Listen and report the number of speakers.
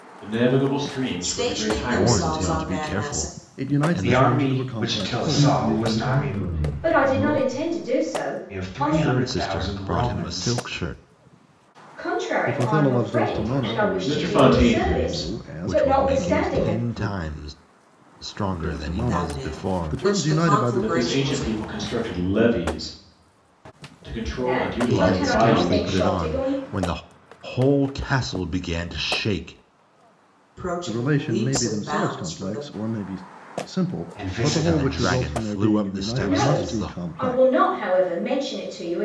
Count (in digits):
7